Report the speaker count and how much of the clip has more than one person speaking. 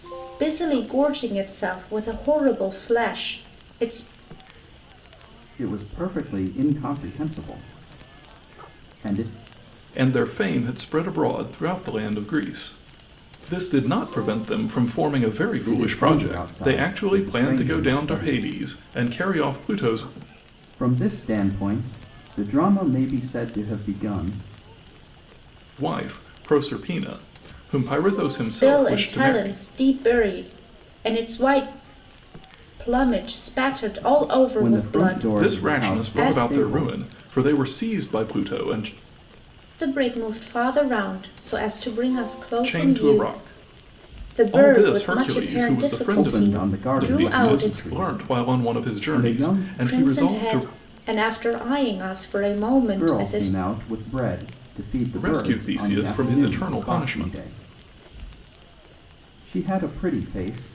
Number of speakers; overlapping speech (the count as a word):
three, about 27%